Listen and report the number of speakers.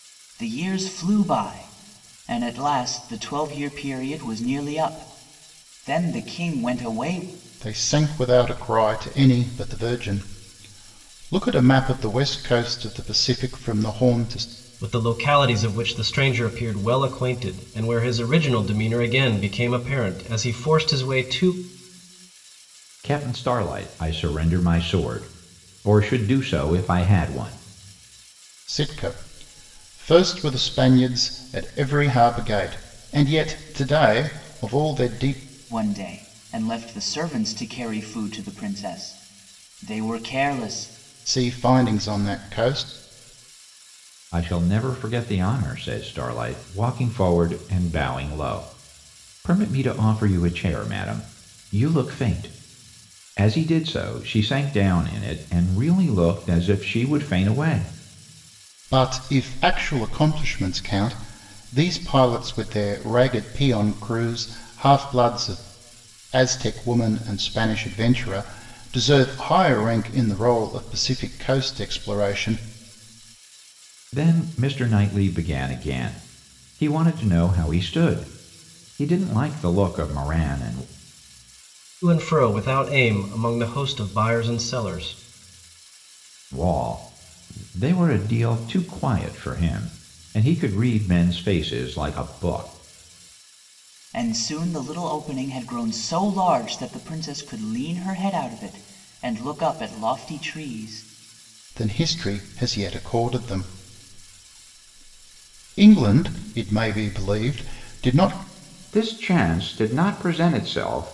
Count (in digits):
4